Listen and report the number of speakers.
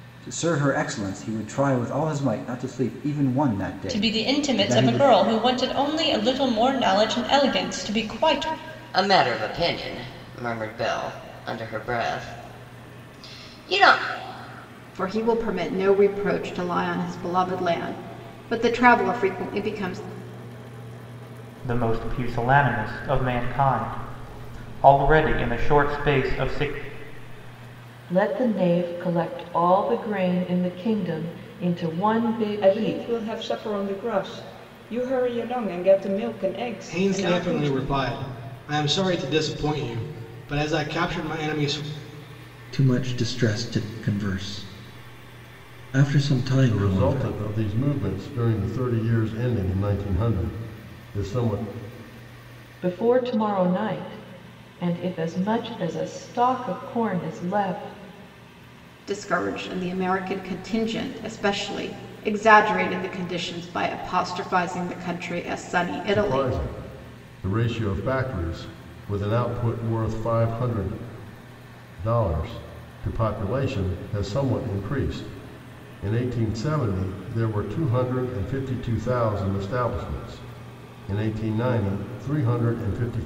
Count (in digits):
10